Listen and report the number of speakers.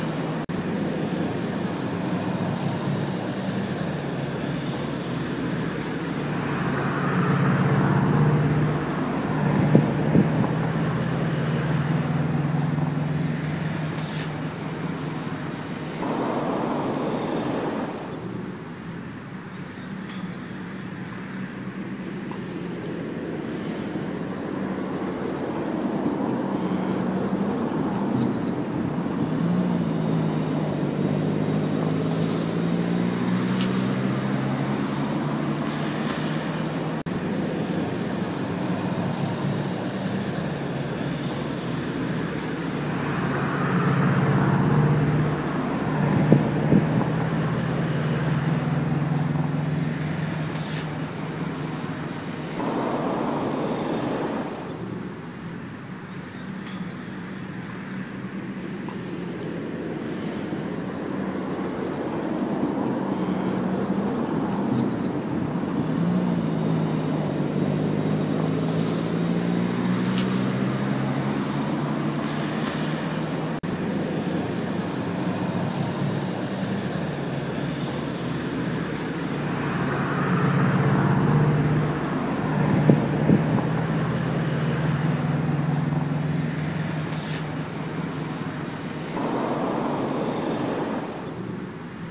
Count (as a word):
zero